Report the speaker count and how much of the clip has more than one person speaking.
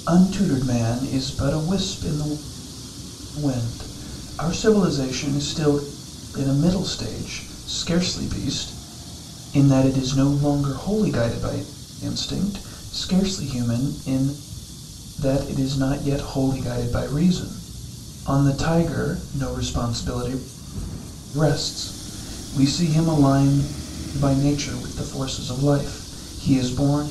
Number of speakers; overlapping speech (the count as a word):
one, no overlap